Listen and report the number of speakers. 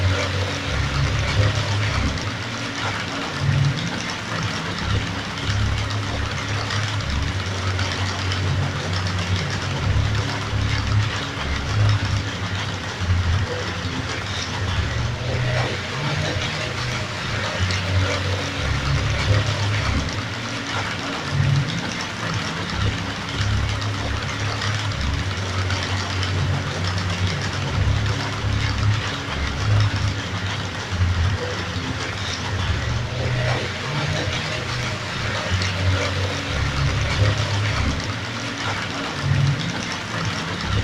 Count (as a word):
zero